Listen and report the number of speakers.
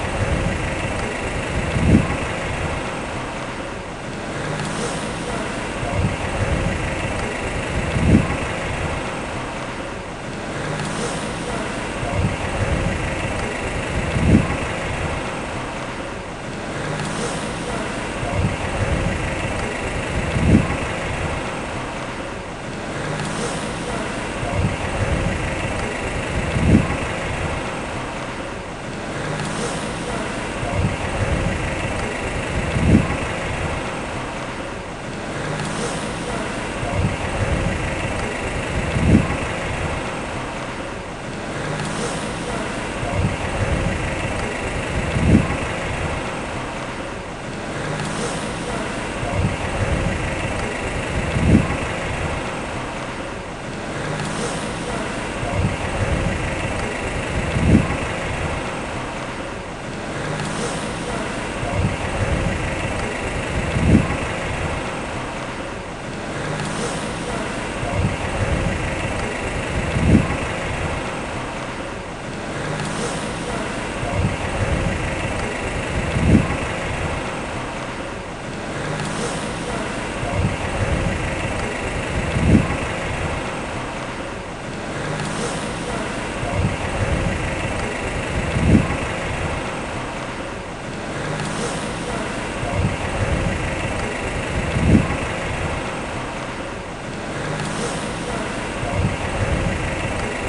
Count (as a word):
zero